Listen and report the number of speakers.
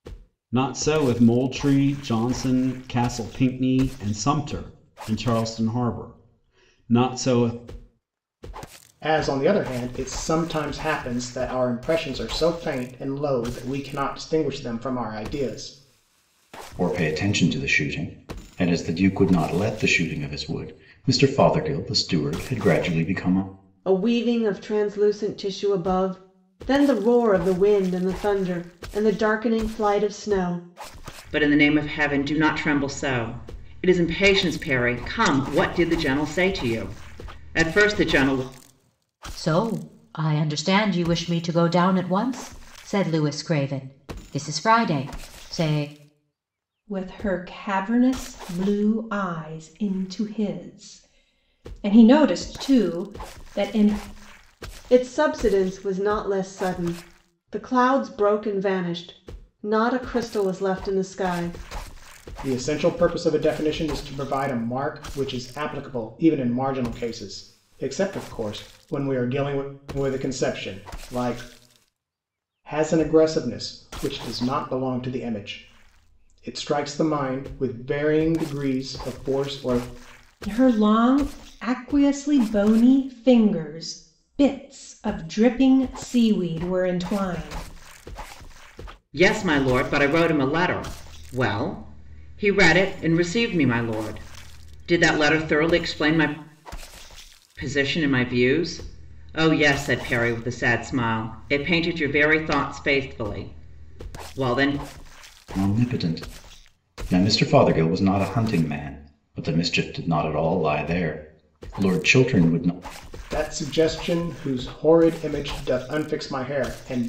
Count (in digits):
7